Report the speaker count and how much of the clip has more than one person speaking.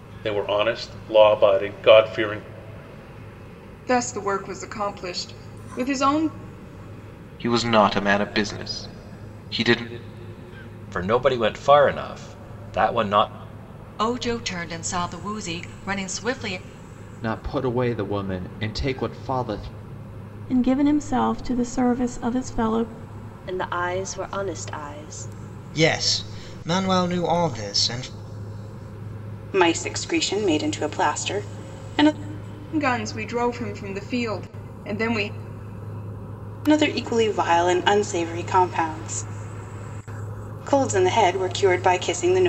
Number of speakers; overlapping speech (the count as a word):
ten, no overlap